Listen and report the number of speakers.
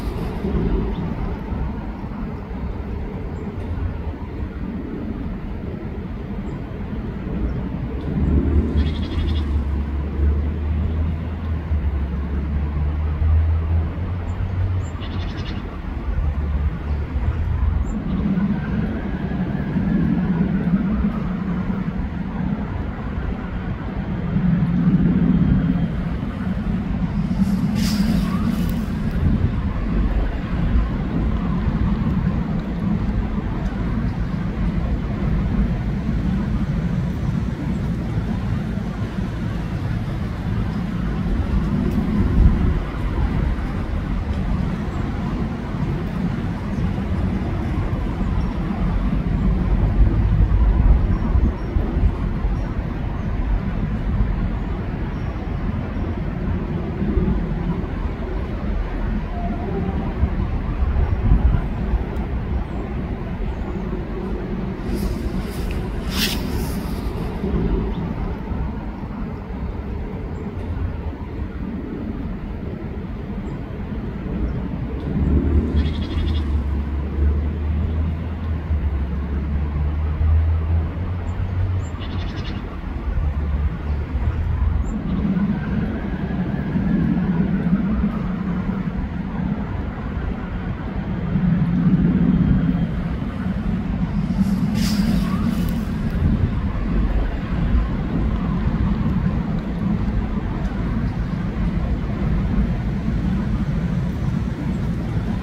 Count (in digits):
0